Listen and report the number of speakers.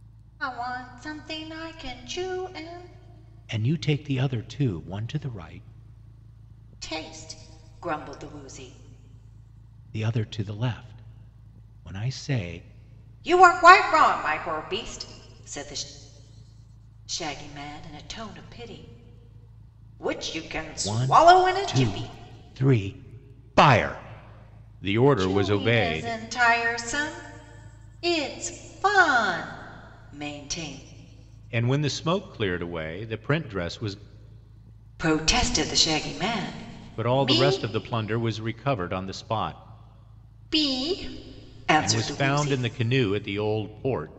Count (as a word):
two